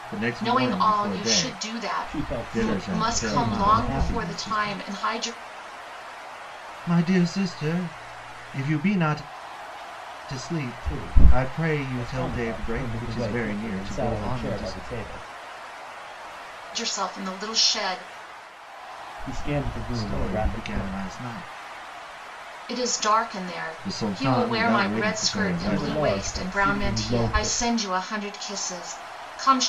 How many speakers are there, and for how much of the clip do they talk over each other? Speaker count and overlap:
three, about 45%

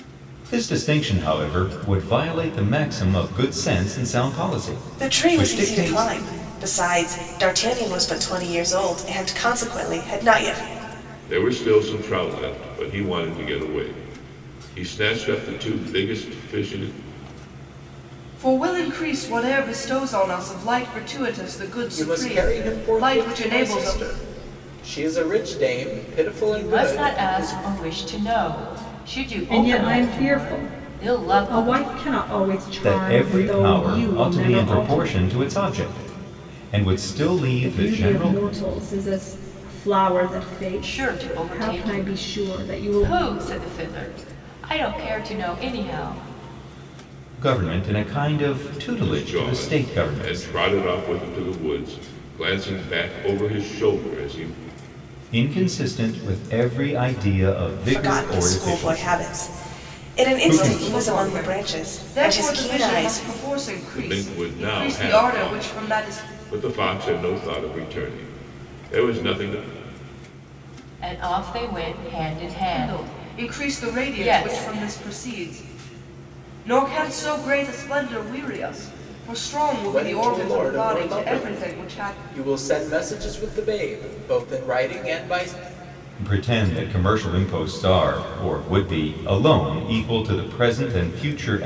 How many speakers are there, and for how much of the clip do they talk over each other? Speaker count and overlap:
seven, about 29%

